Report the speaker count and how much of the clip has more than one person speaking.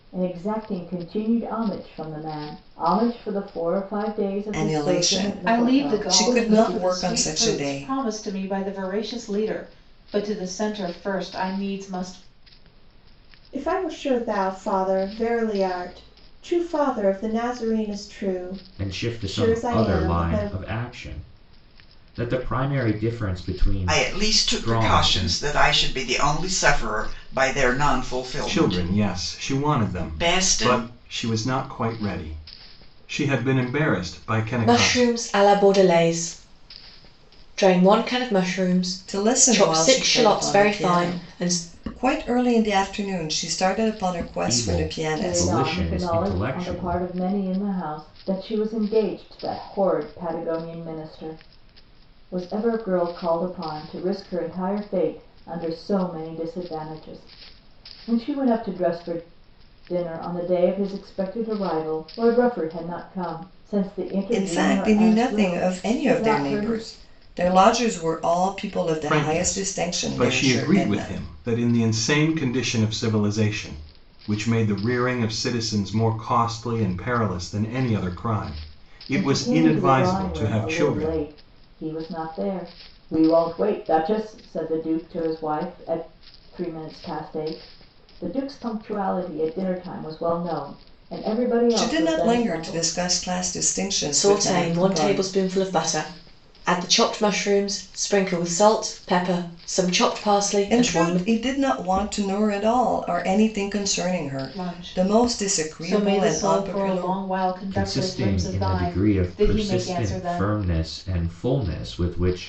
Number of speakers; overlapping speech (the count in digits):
8, about 27%